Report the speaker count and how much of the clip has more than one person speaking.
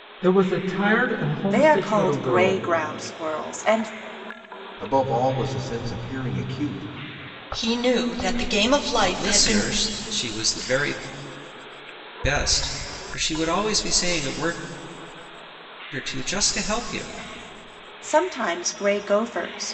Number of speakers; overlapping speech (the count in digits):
5, about 9%